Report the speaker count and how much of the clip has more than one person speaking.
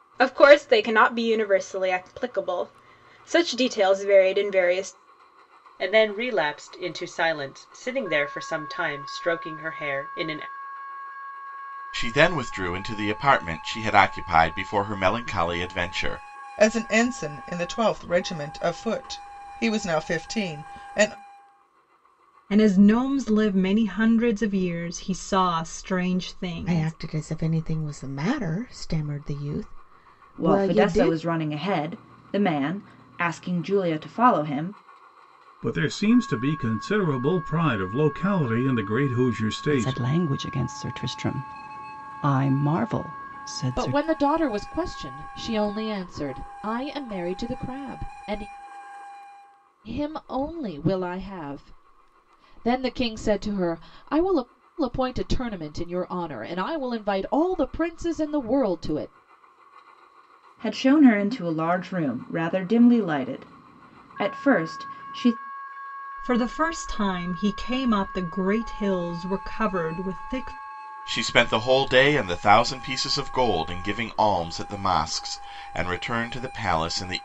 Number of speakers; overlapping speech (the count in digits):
10, about 2%